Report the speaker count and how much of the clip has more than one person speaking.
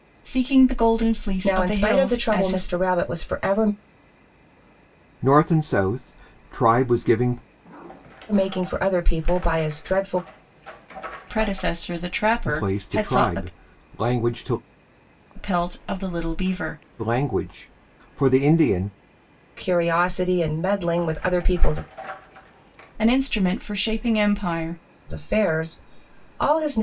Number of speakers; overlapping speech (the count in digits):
3, about 9%